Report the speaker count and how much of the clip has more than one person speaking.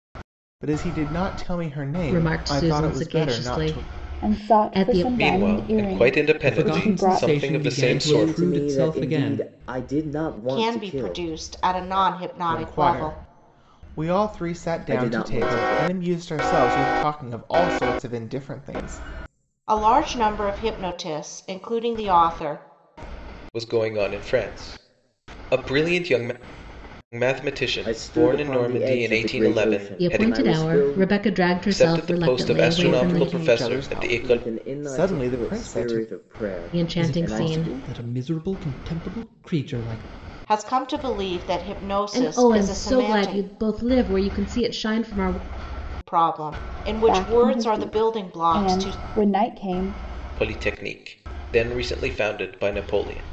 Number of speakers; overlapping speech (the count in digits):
7, about 41%